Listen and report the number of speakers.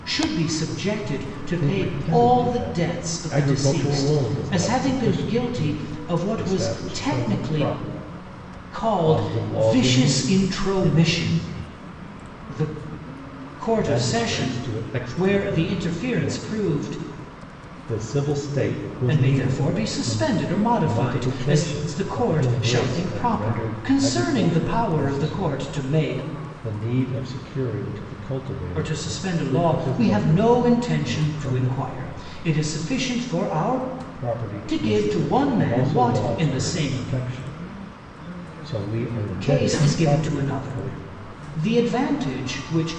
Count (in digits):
2